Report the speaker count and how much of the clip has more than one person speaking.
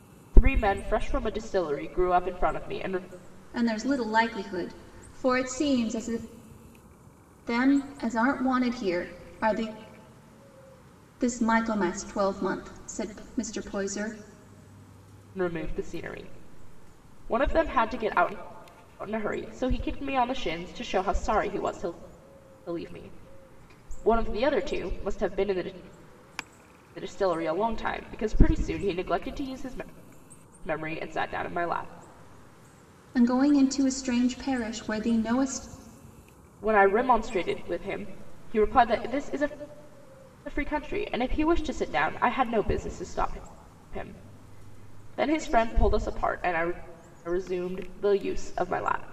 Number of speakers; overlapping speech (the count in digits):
2, no overlap